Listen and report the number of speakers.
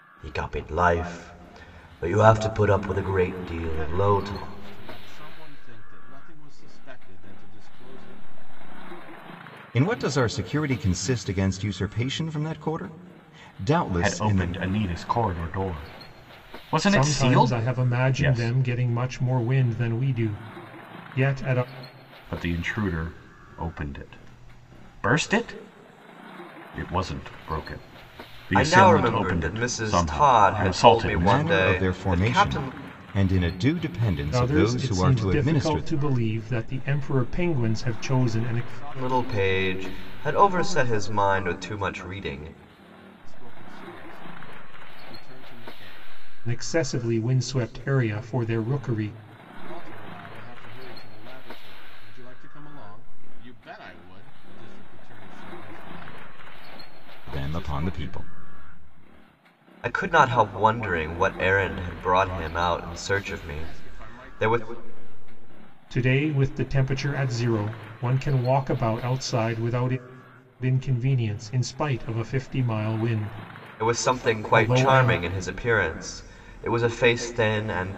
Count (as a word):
five